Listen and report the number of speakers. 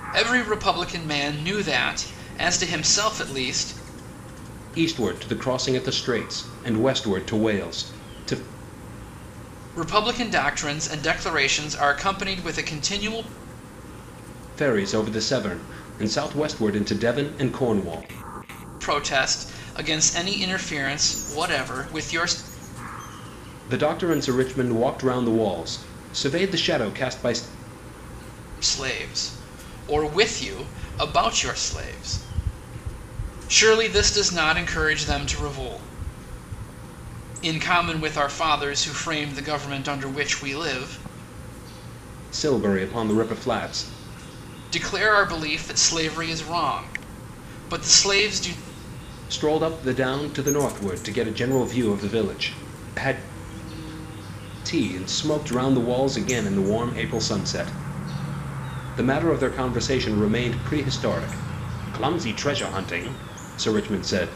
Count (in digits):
2